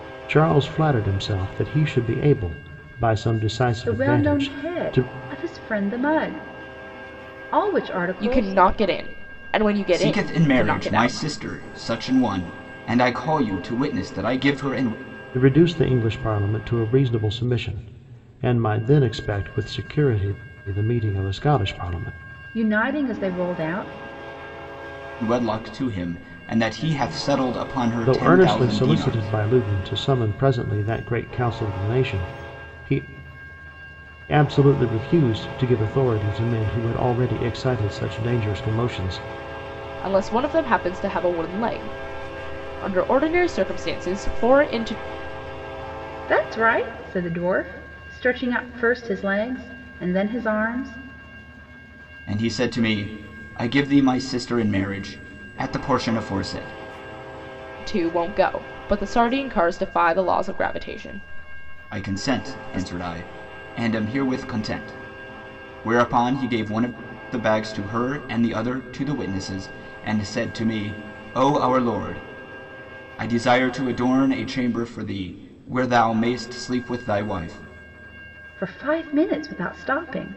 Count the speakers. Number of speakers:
4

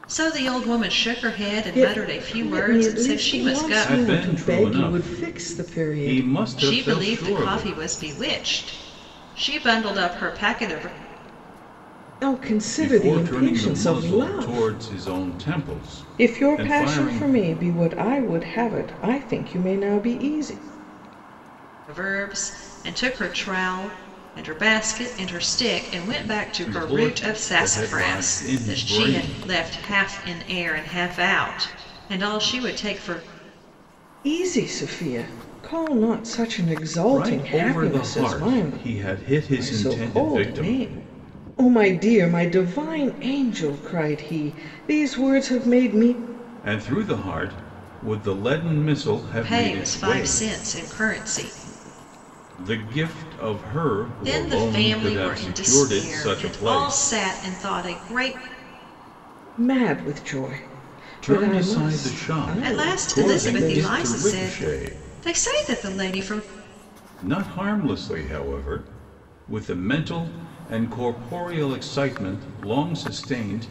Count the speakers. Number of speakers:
3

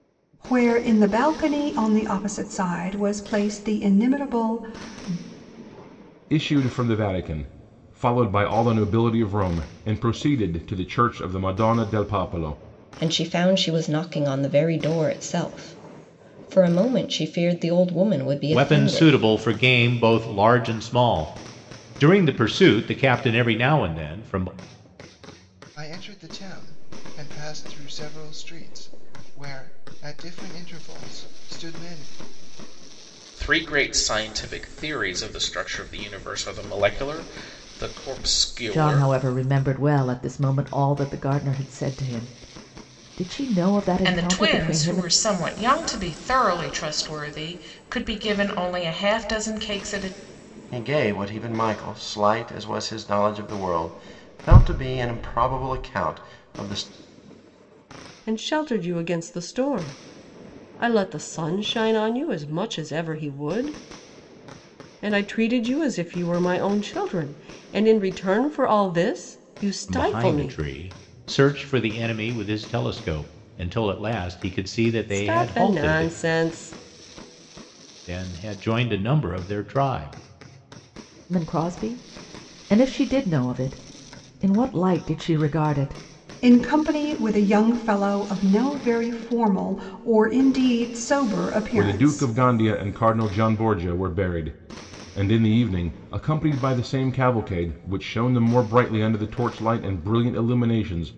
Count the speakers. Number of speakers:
10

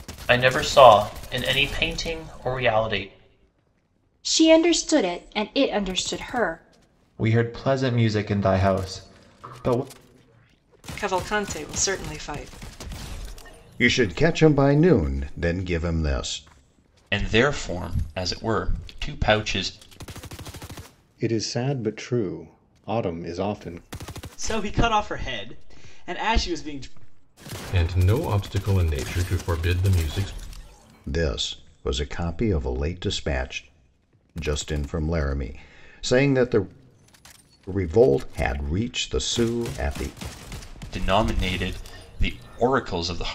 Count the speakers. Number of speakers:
9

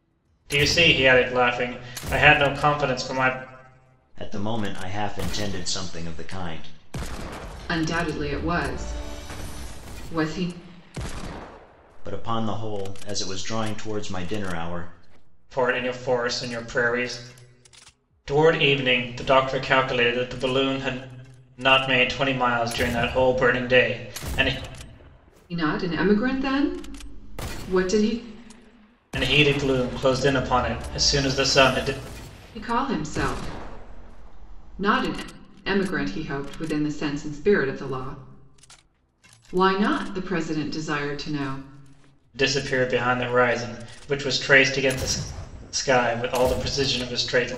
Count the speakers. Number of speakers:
3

